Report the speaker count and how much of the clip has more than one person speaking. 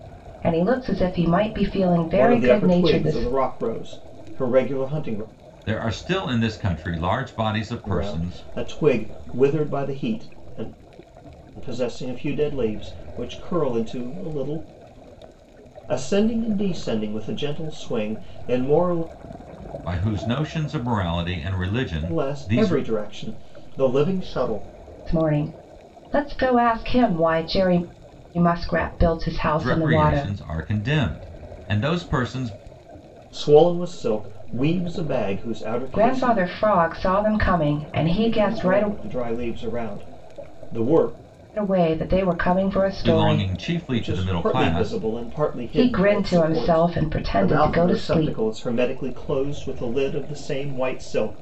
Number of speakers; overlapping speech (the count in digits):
3, about 16%